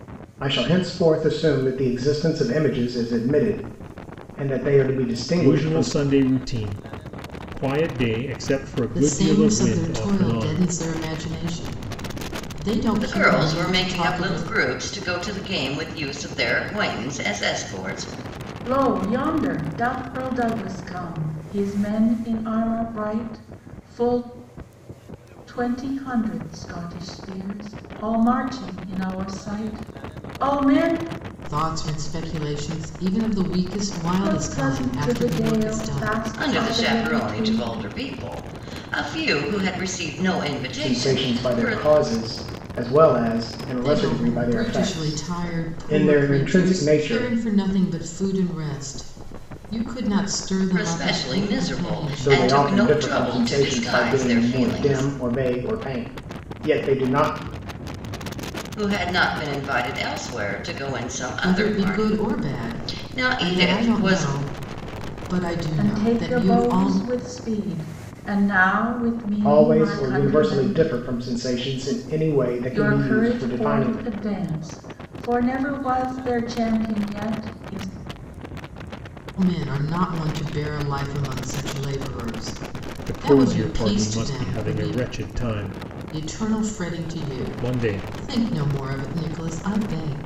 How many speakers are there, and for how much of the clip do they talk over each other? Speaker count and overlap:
5, about 30%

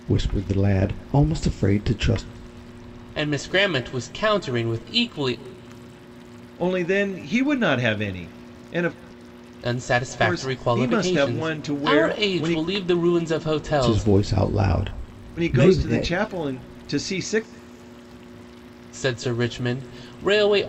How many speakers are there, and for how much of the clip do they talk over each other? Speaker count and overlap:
3, about 16%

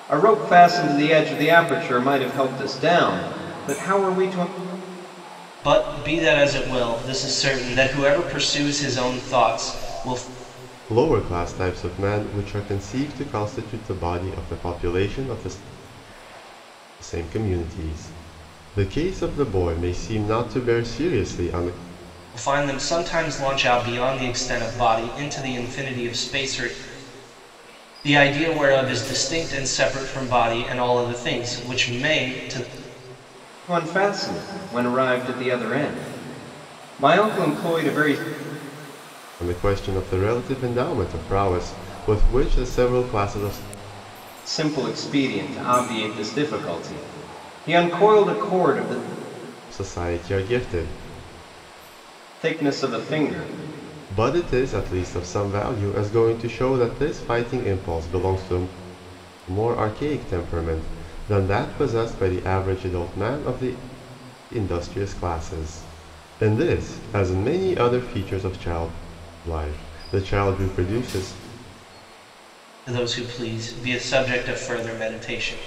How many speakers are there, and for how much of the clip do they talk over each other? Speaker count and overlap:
3, no overlap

